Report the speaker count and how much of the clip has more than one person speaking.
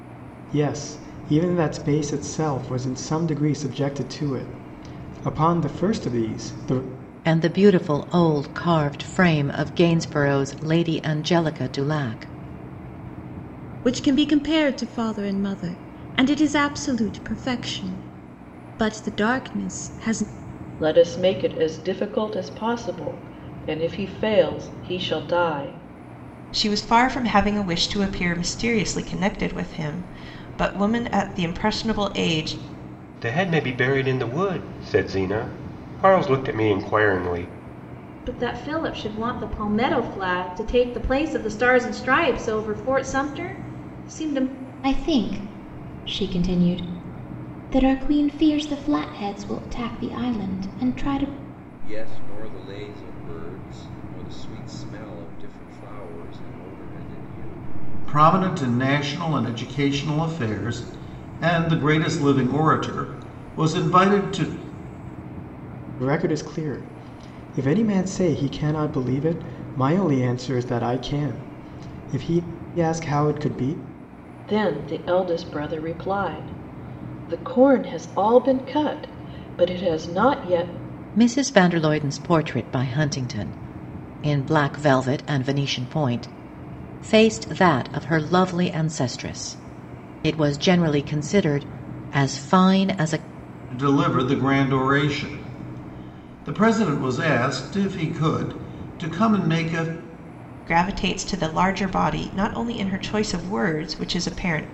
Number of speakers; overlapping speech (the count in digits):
10, no overlap